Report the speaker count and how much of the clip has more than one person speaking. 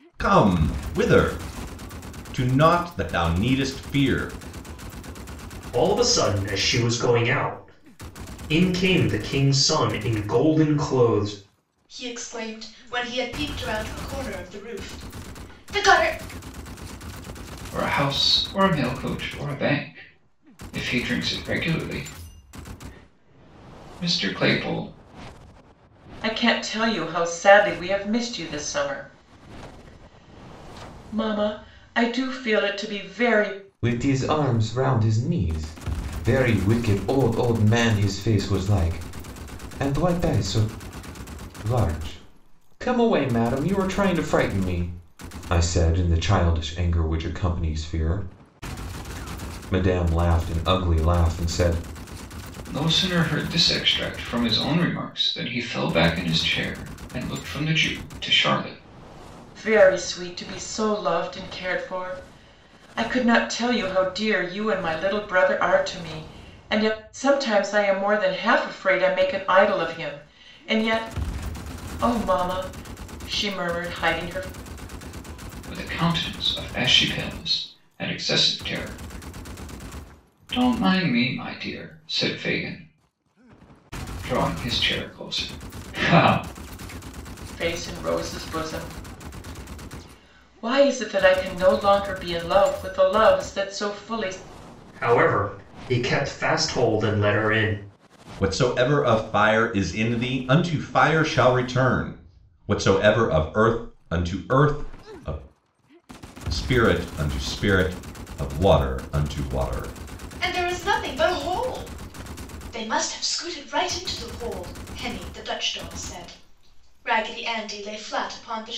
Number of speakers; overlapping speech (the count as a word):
six, no overlap